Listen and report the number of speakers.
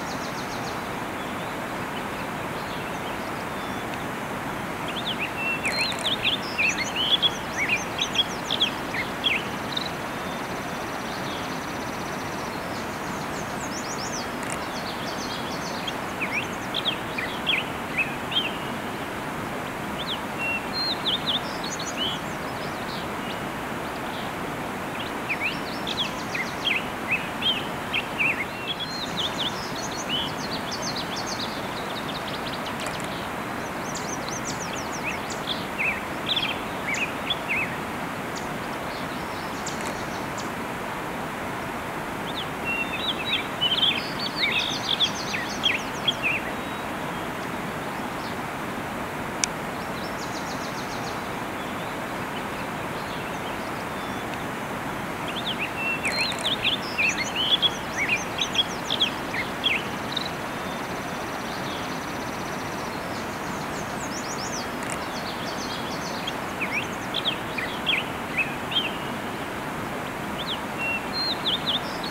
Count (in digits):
0